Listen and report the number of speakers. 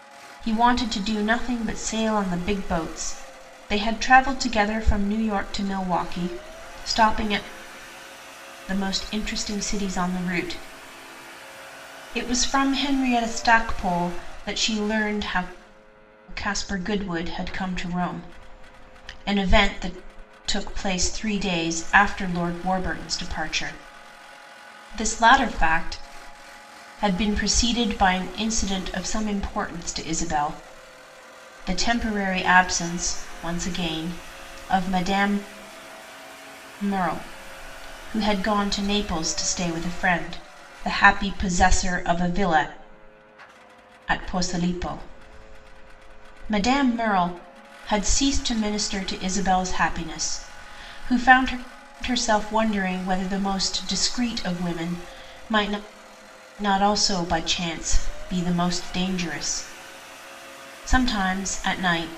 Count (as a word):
one